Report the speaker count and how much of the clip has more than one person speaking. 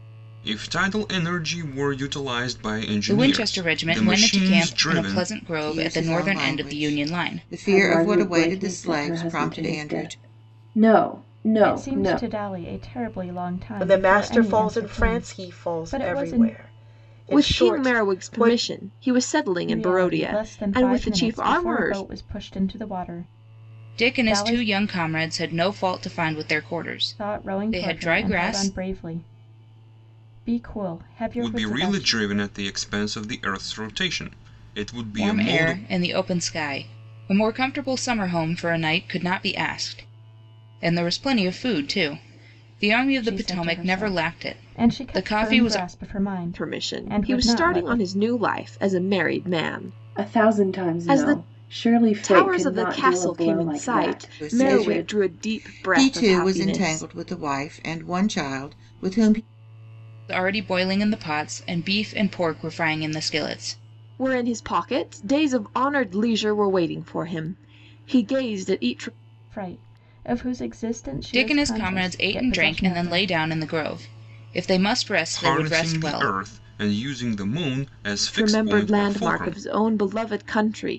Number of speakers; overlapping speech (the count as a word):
seven, about 40%